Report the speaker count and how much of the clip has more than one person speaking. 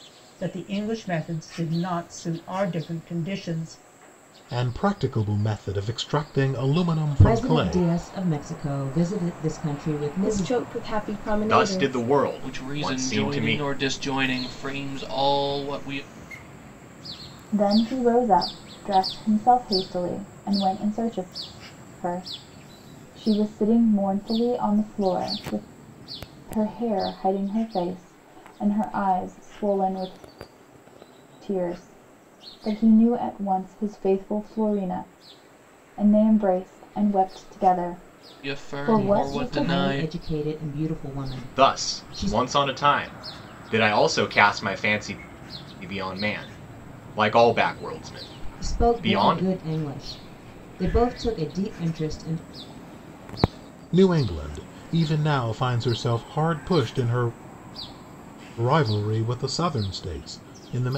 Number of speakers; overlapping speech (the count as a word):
seven, about 10%